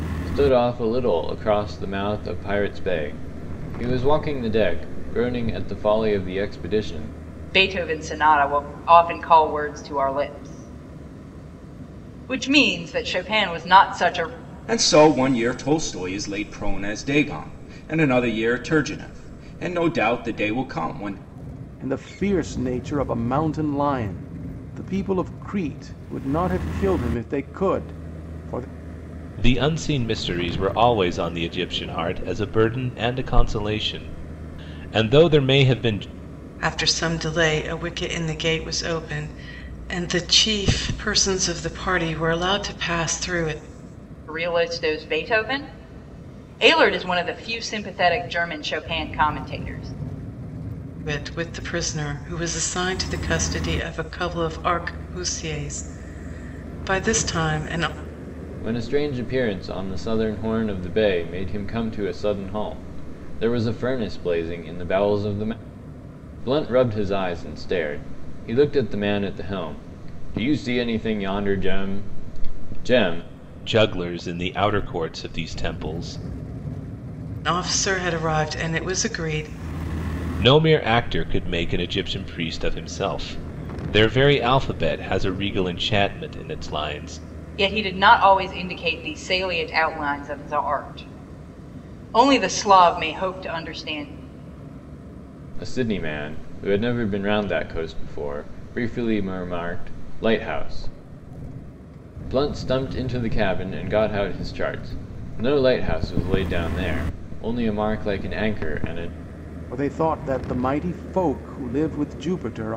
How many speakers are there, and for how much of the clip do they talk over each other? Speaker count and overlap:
6, no overlap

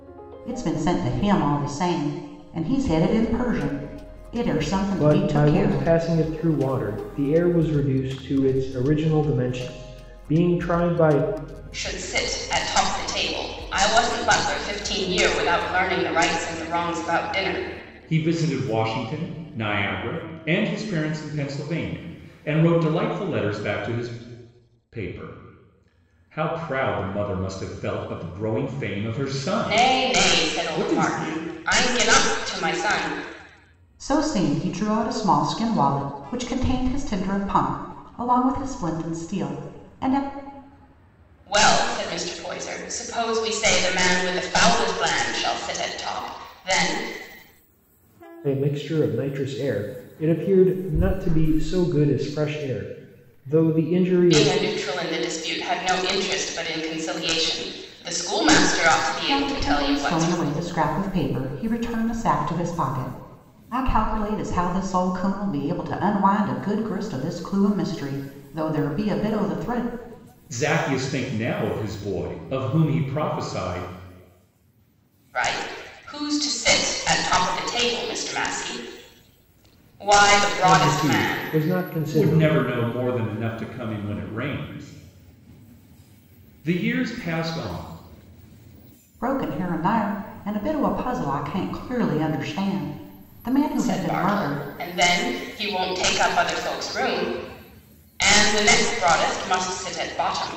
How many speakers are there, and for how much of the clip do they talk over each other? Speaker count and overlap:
4, about 6%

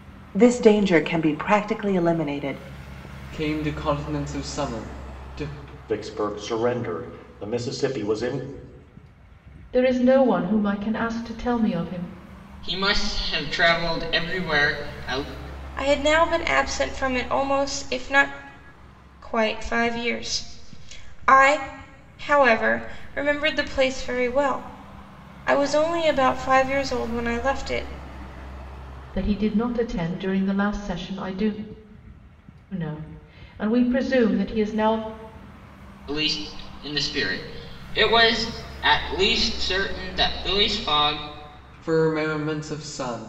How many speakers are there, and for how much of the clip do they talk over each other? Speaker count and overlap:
6, no overlap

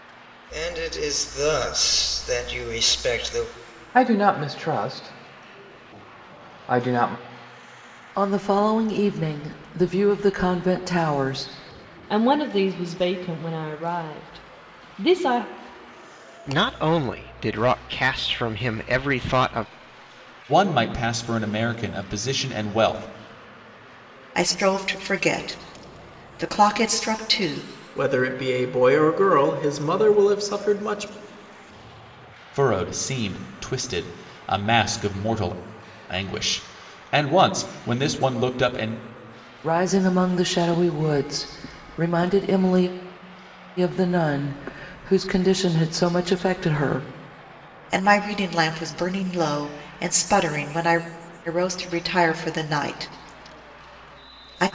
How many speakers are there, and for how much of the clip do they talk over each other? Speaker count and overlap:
8, no overlap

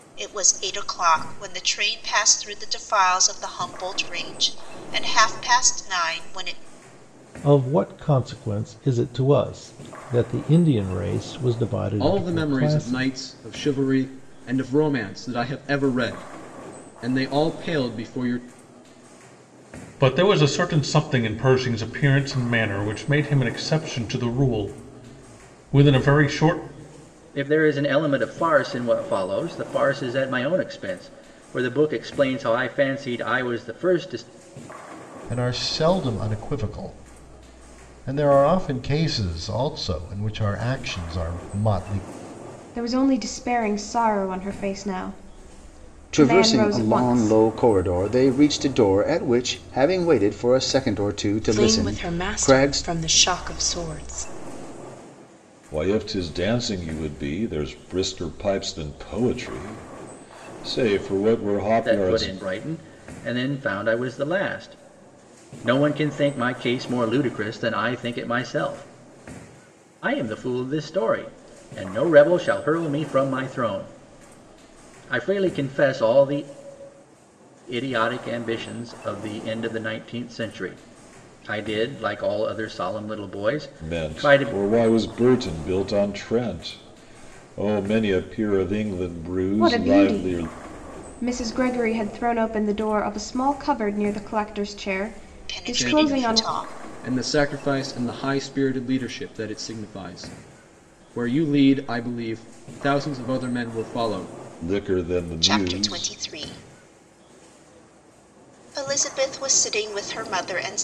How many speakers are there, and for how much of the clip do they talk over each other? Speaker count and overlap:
10, about 8%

